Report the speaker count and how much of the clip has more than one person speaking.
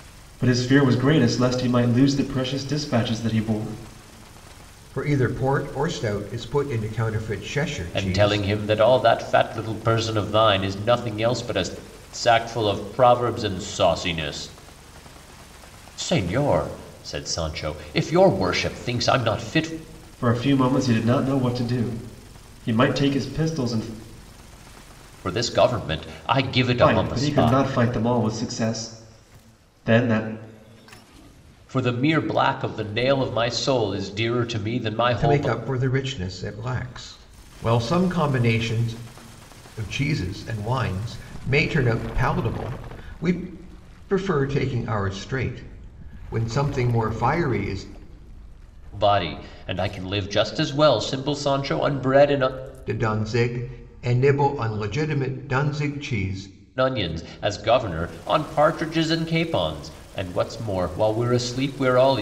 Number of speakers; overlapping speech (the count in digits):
3, about 3%